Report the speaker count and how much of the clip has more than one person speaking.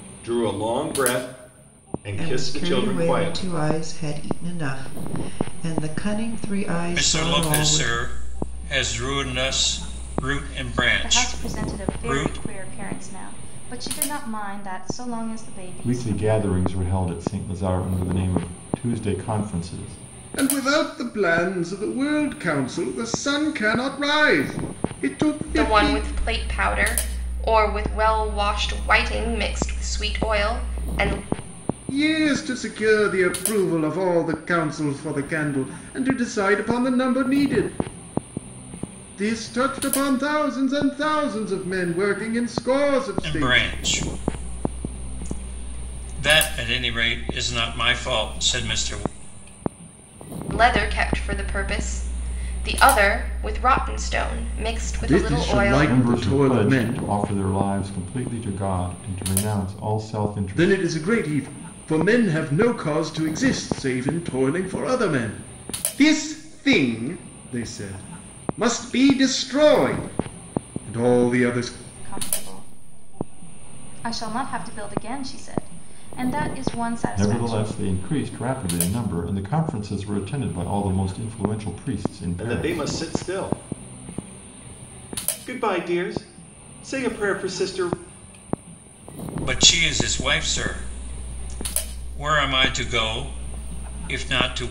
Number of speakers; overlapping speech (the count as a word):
seven, about 10%